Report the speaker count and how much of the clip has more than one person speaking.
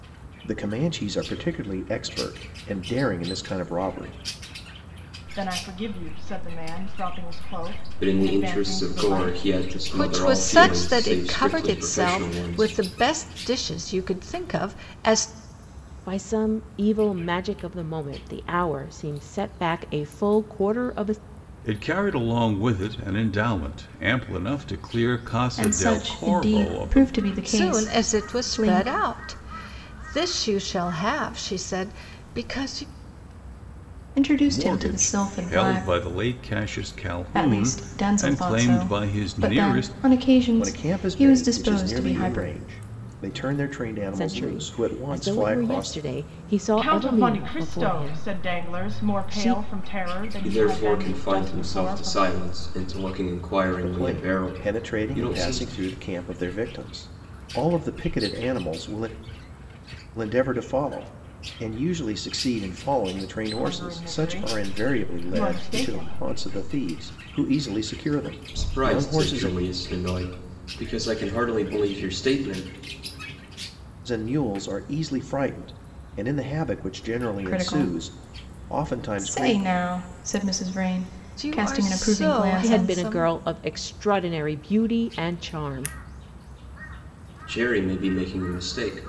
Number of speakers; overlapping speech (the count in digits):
7, about 34%